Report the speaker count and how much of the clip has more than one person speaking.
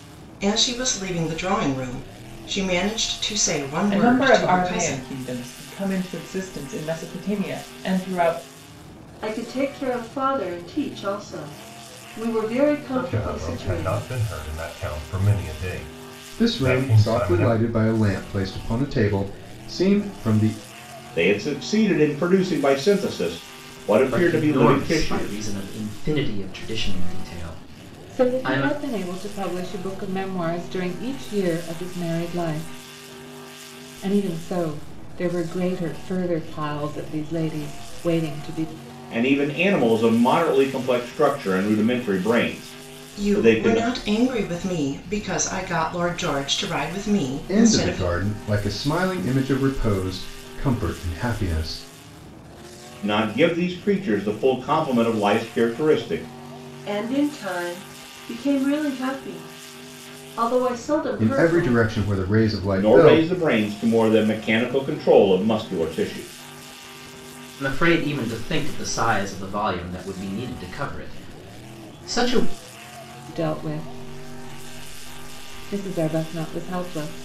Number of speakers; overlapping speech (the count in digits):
8, about 10%